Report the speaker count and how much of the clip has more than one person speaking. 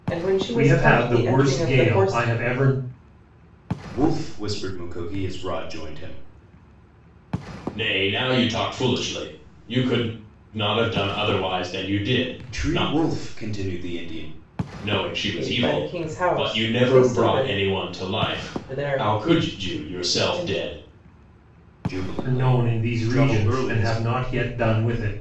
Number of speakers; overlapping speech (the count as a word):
four, about 32%